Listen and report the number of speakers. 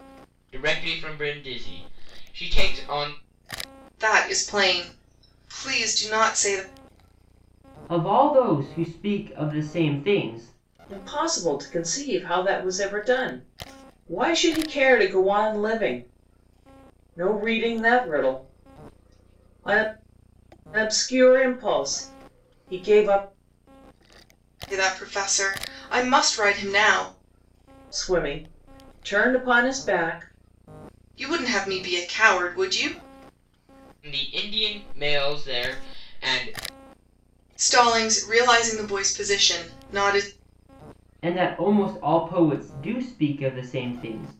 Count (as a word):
four